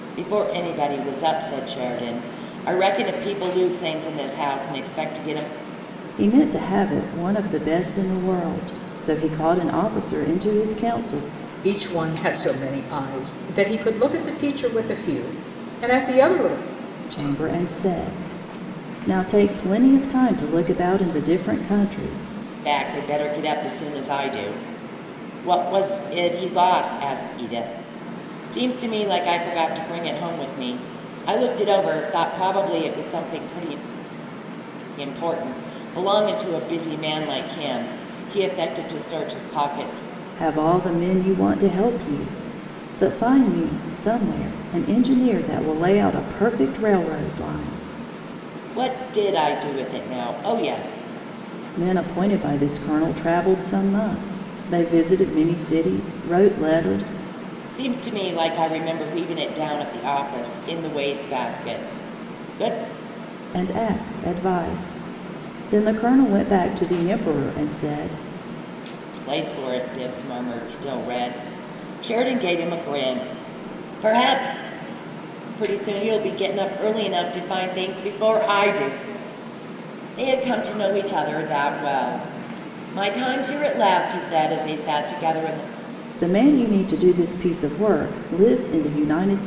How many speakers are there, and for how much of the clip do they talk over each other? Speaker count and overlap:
three, no overlap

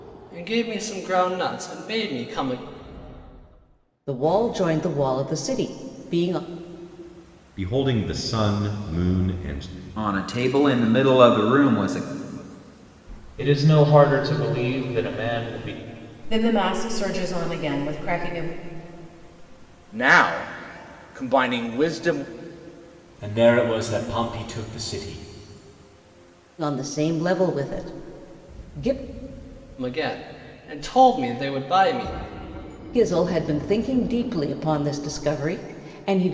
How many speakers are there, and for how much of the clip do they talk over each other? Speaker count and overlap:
eight, no overlap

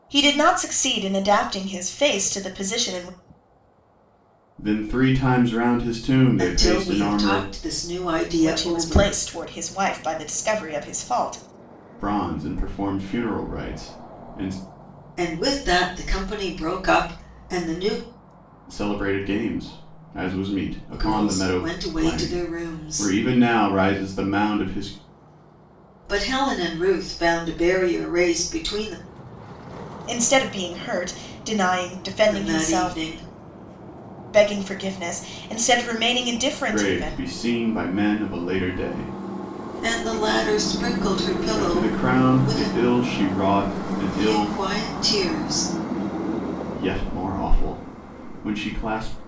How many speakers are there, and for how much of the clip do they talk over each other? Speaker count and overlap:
three, about 14%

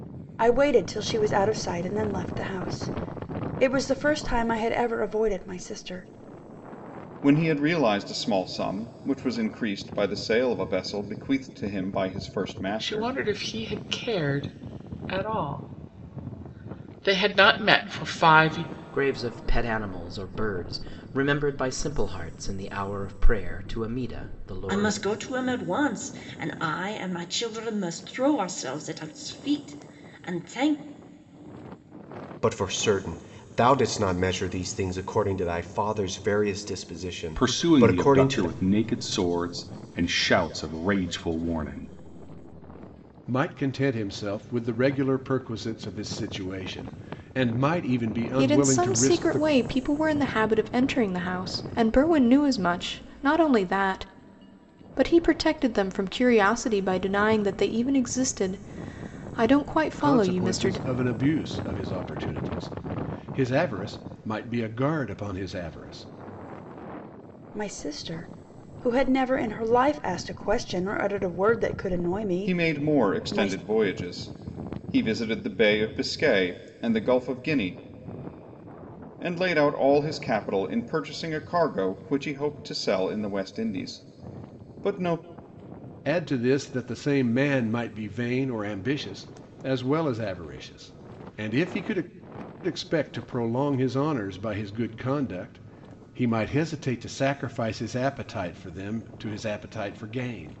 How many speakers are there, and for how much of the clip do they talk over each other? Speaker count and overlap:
nine, about 5%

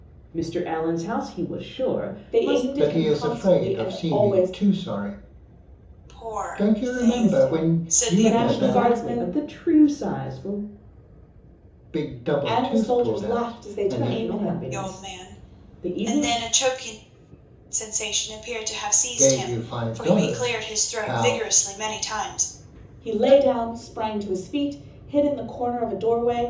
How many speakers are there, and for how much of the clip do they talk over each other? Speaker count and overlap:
four, about 43%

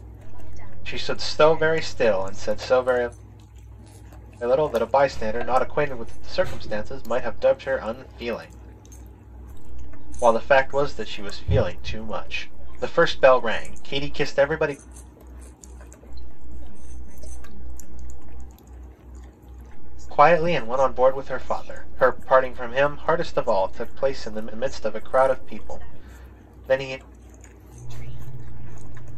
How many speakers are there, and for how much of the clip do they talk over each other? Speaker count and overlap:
two, about 48%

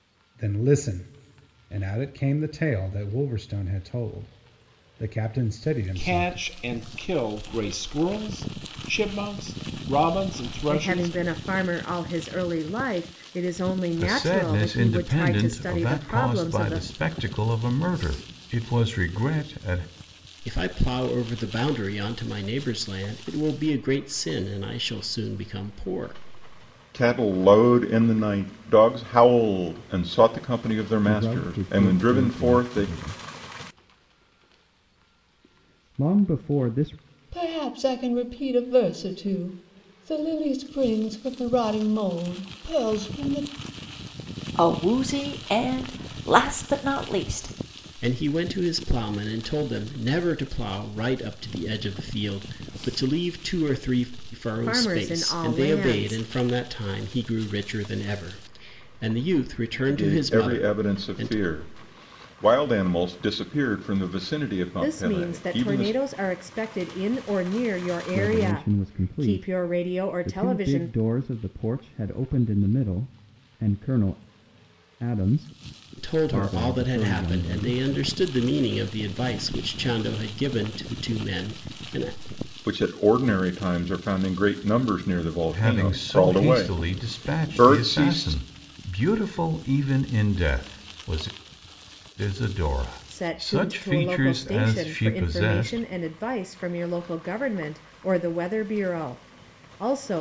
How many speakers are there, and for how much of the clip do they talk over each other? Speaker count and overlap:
nine, about 21%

